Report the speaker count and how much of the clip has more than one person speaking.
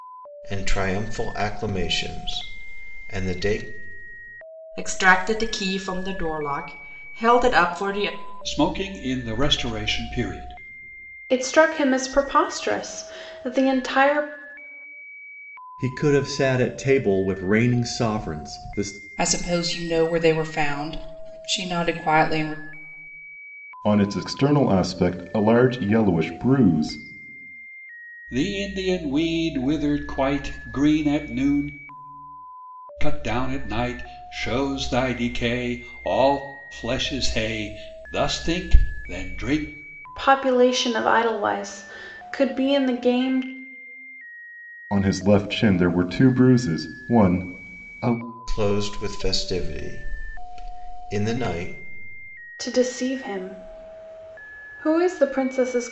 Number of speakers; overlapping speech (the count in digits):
7, no overlap